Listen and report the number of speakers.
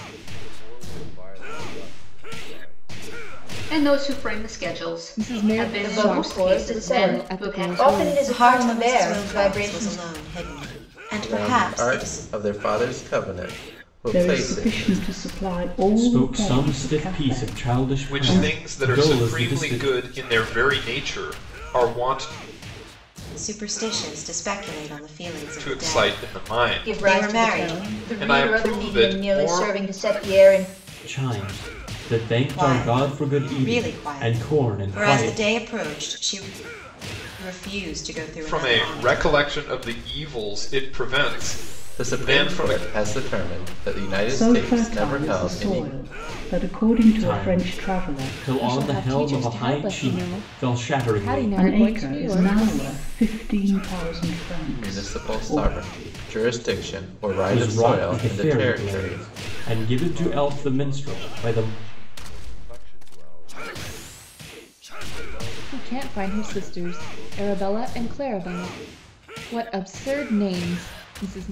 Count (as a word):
nine